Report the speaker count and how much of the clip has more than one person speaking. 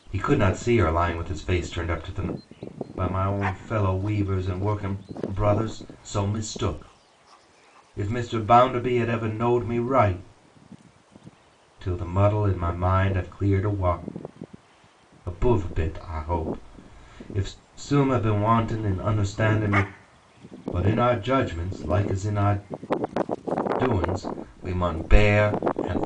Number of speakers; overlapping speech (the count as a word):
one, no overlap